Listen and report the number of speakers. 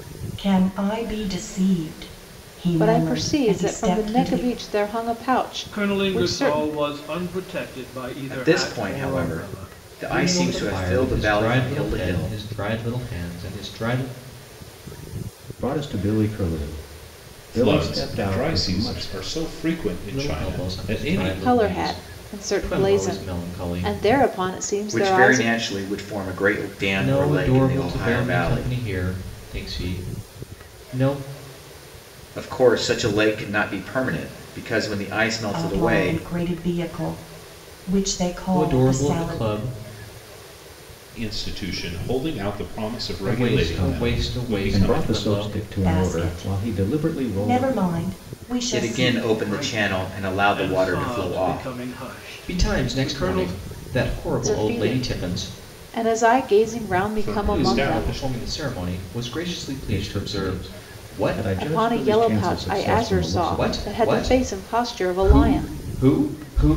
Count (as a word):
seven